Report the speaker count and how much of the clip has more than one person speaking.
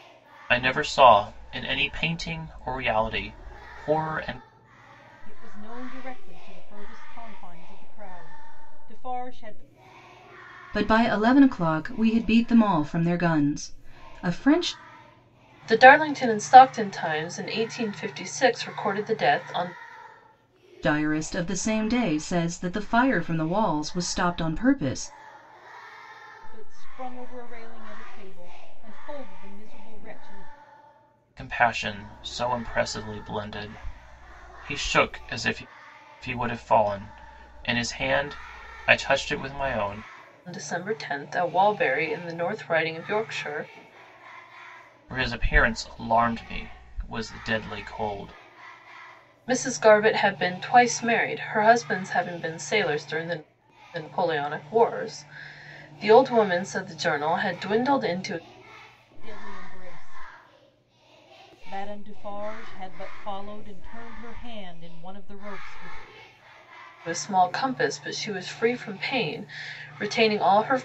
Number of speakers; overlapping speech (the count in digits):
4, no overlap